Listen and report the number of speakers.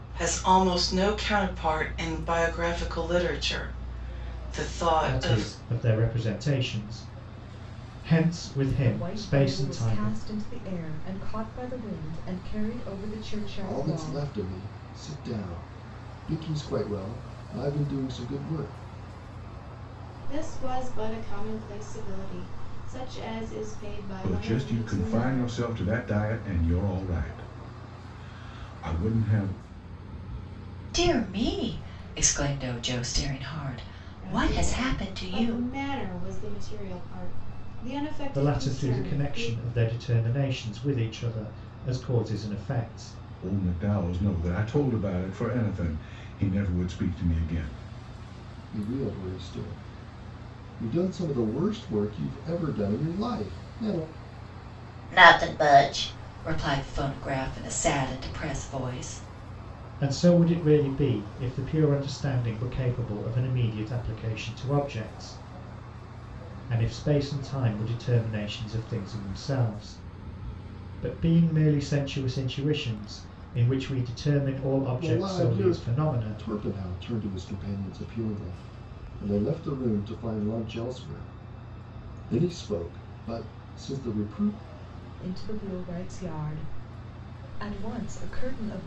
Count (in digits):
7